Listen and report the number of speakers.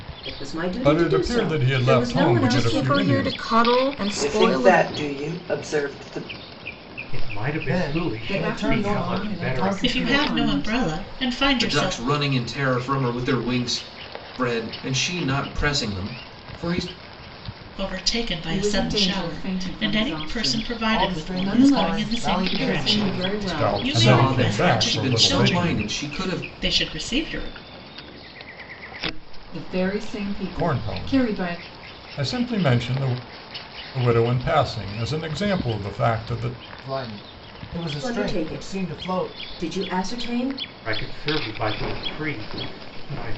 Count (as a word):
nine